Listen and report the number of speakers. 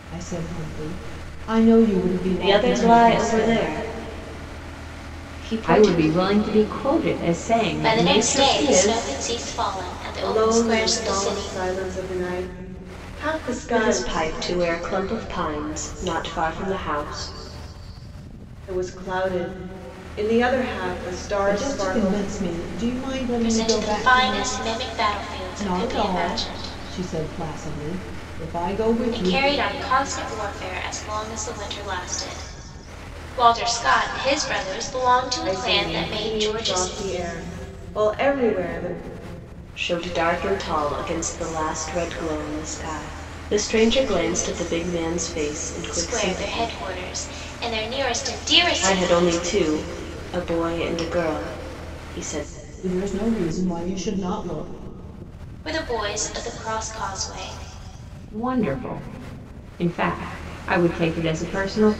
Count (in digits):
5